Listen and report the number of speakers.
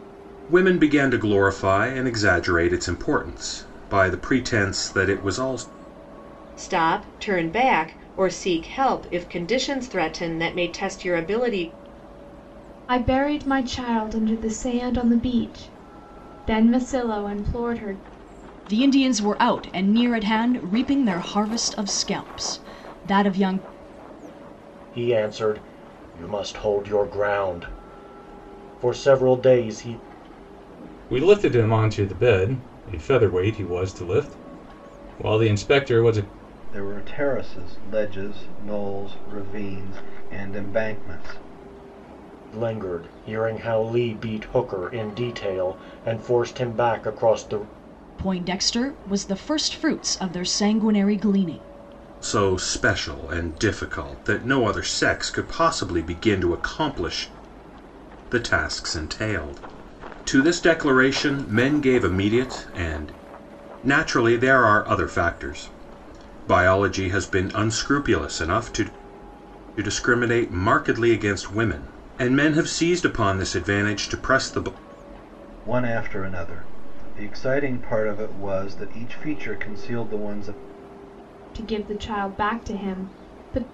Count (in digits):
7